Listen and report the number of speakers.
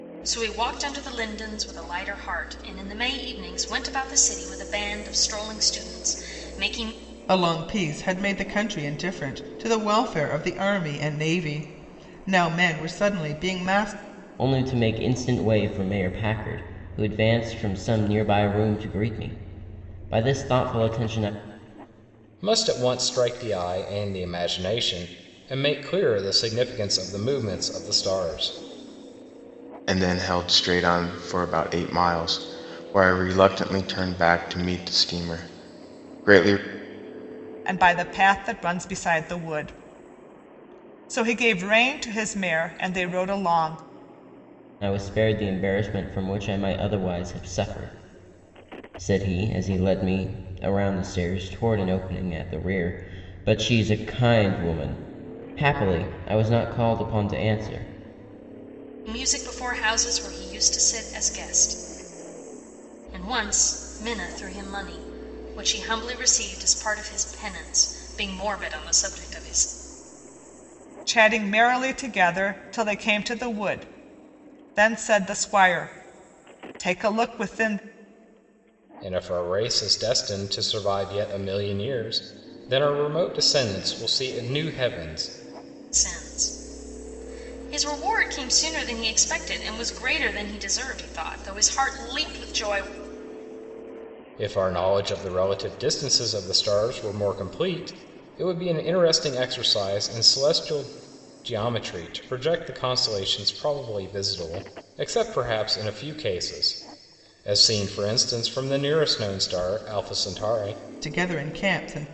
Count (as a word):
six